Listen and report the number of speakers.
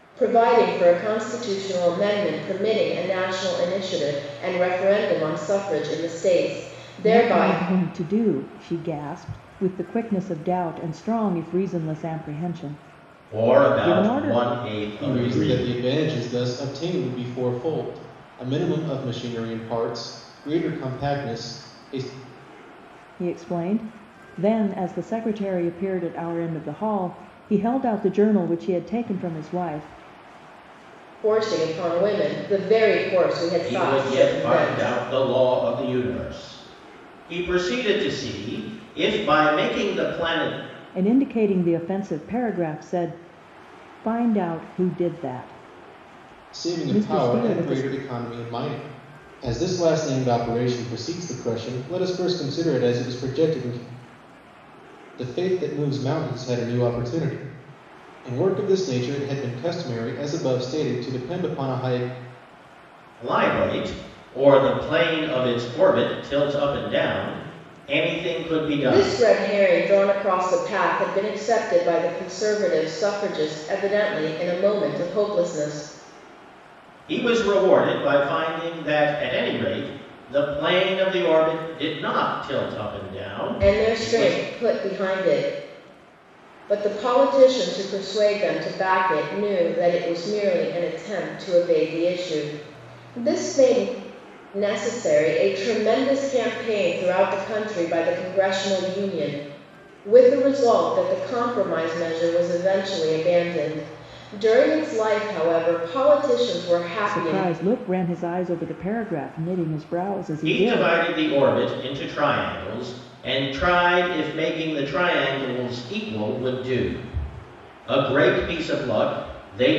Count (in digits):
4